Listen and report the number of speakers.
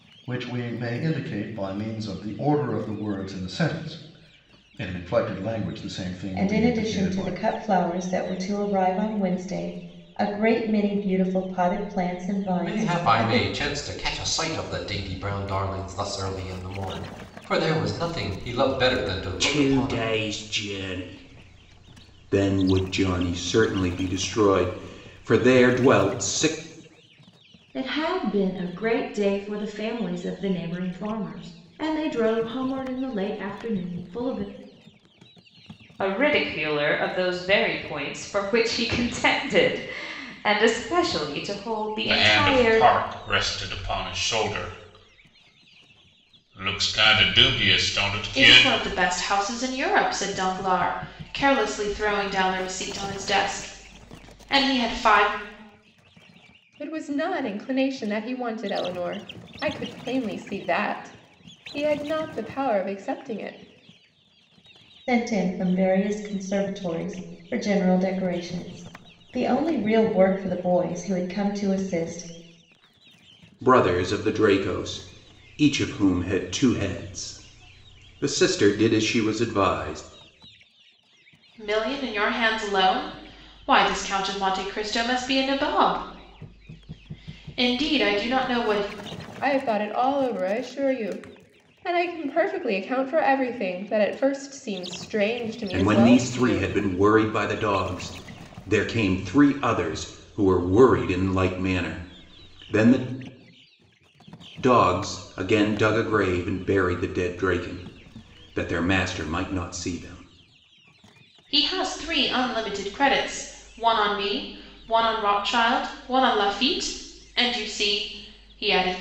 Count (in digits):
9